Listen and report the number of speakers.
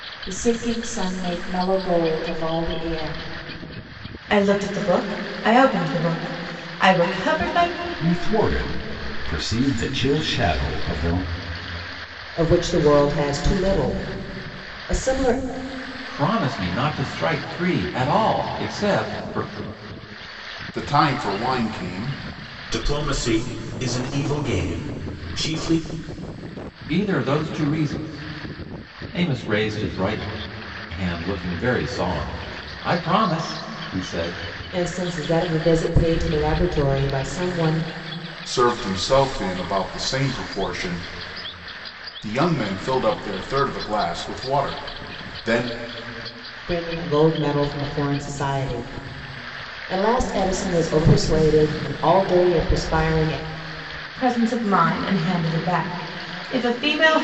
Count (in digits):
7